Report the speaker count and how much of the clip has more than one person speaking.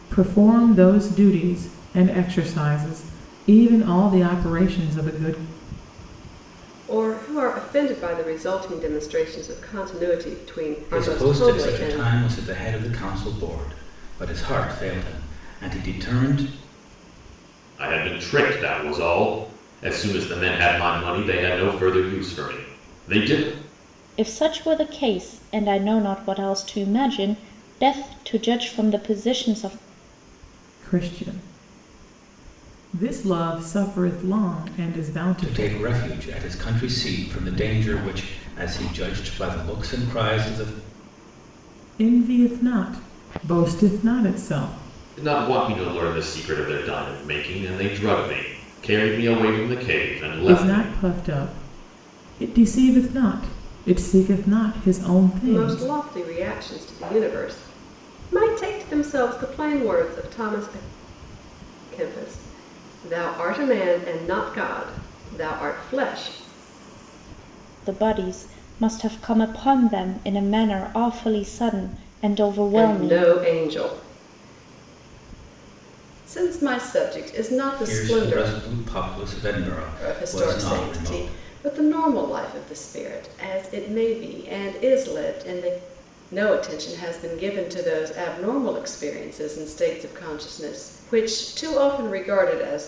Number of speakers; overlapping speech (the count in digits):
5, about 6%